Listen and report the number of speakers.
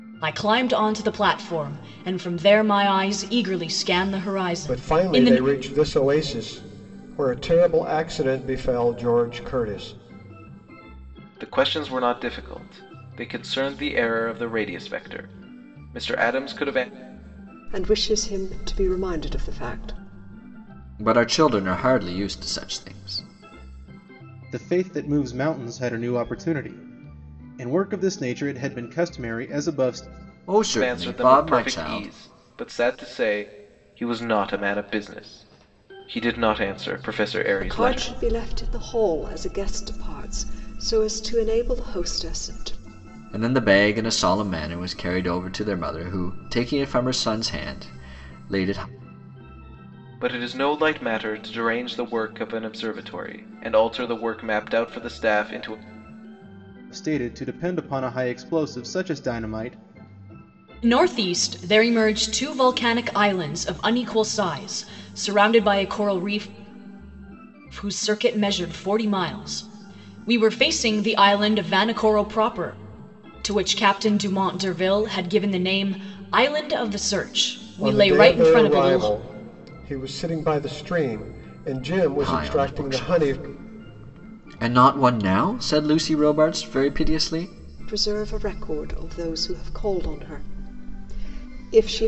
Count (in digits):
6